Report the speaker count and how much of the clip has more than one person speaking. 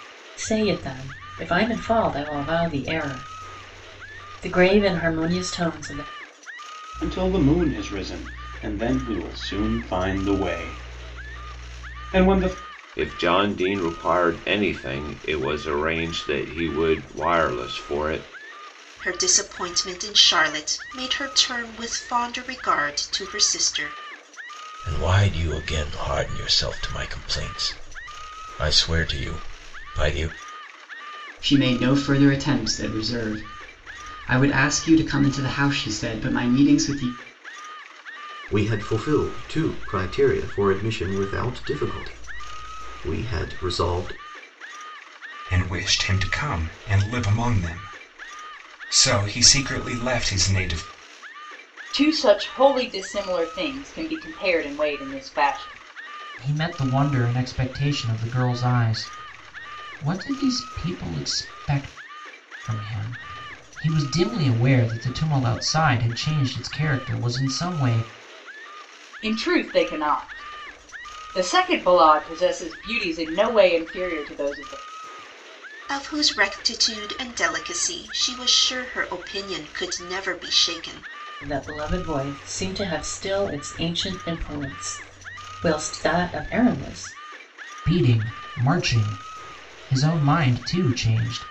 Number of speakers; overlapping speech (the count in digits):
10, no overlap